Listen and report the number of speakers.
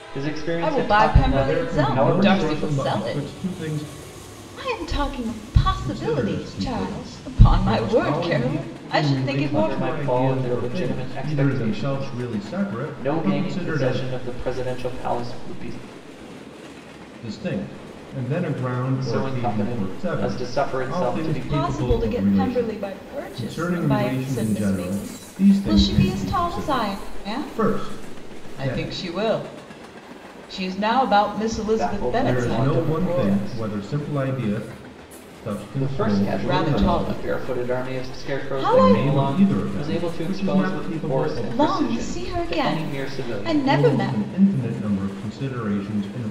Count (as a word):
three